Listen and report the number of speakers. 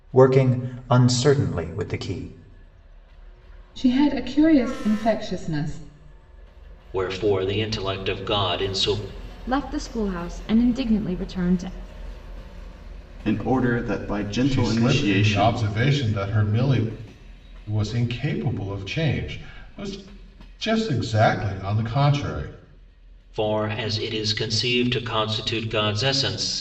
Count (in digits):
6